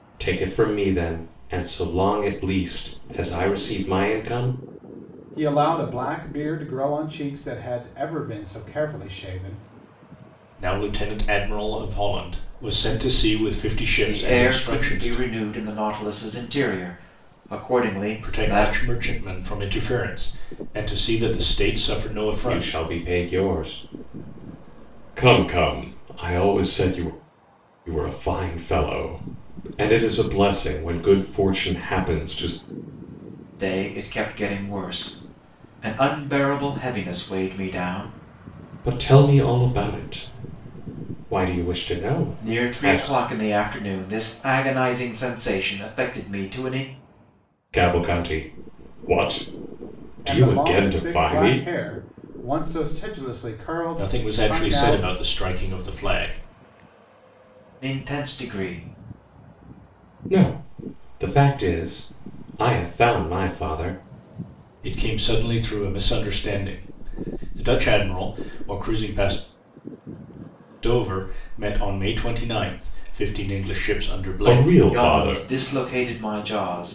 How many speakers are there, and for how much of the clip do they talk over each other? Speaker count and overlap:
4, about 9%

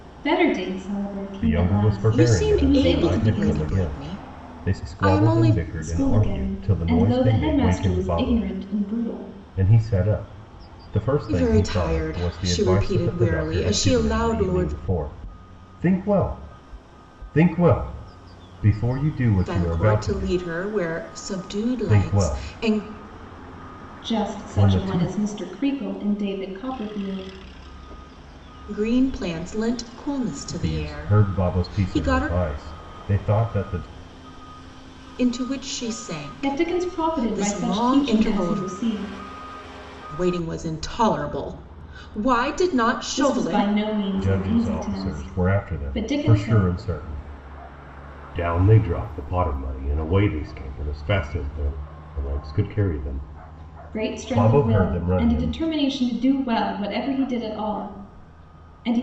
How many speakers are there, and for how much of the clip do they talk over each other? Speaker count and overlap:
3, about 38%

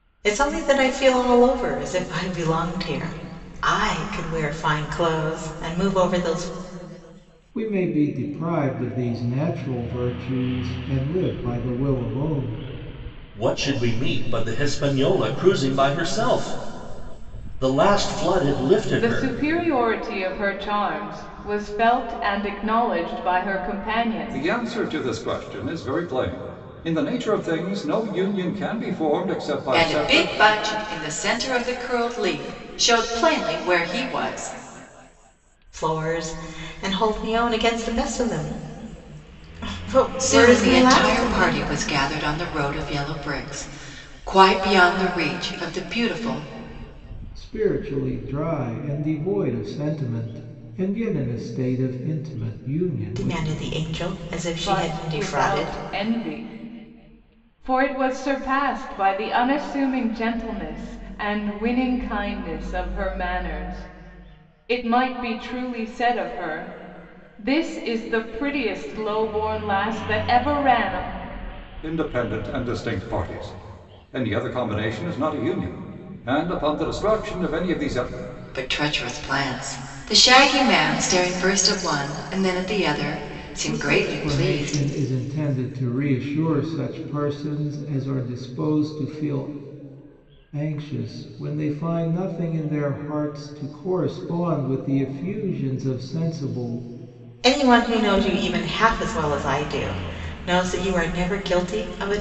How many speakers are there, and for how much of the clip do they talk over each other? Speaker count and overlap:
6, about 6%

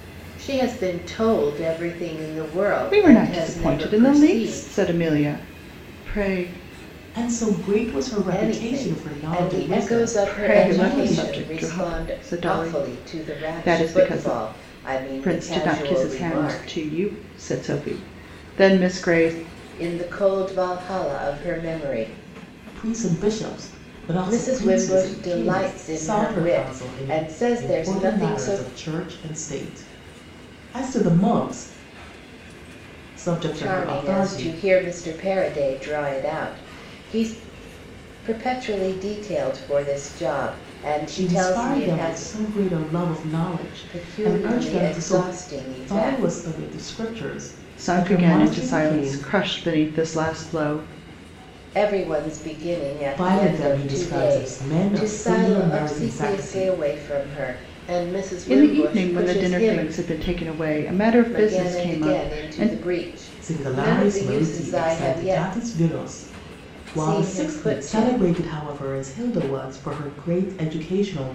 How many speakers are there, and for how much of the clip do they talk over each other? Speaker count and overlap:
3, about 41%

